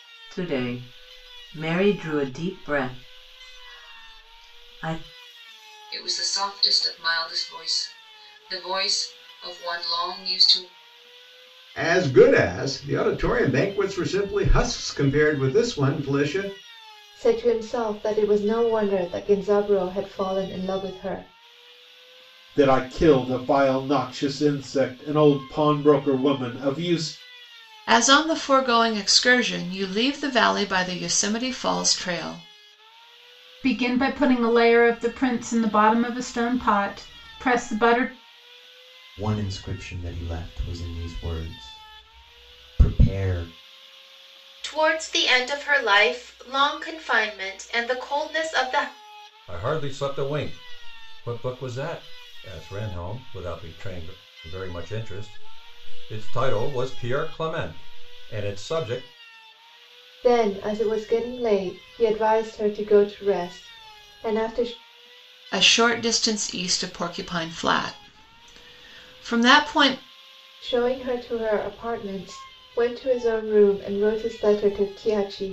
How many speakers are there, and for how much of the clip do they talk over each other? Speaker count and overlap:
ten, no overlap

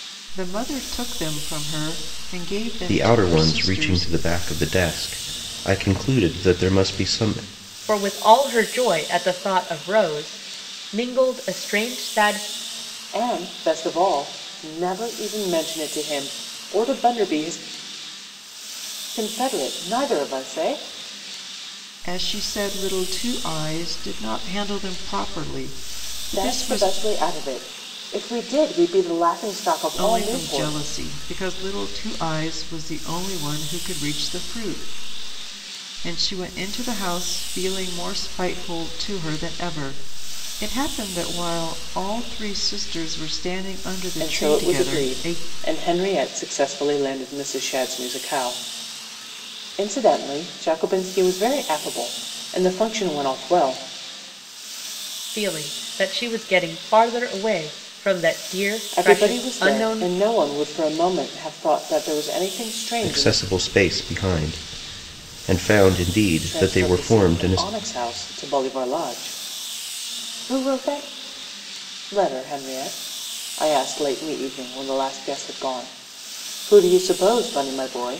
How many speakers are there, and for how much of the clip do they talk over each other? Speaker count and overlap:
four, about 9%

